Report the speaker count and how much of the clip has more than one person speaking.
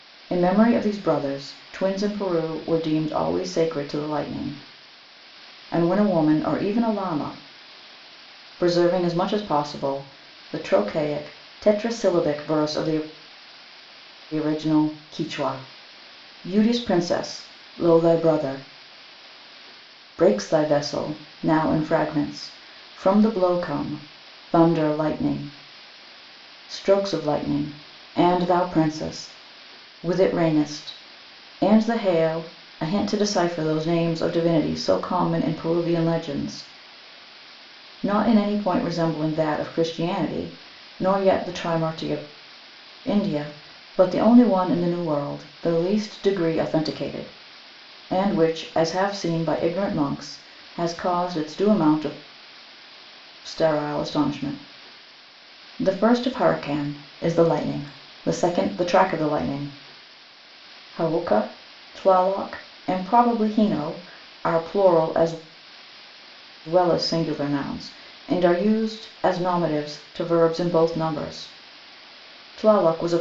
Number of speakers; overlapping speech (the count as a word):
one, no overlap